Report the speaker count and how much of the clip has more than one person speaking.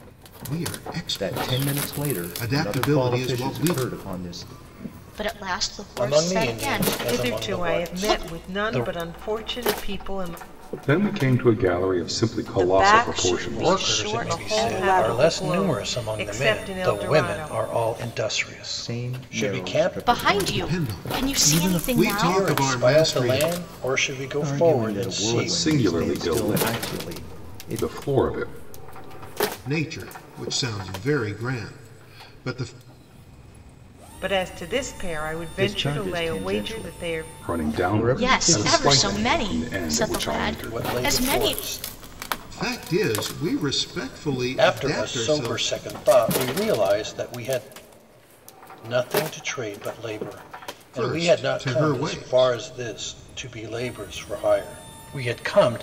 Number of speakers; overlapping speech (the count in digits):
7, about 50%